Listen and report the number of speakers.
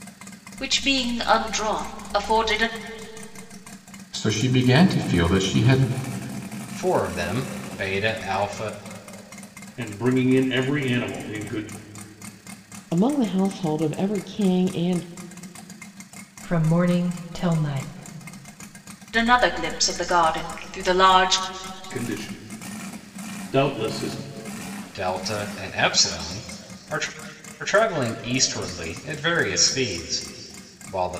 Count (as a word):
six